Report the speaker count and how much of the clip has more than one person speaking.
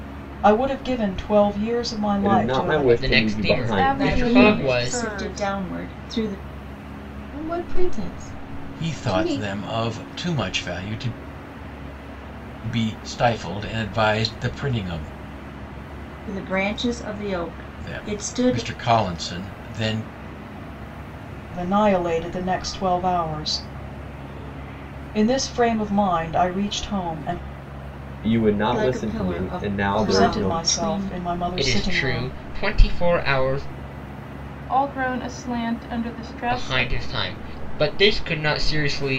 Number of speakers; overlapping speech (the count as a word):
seven, about 22%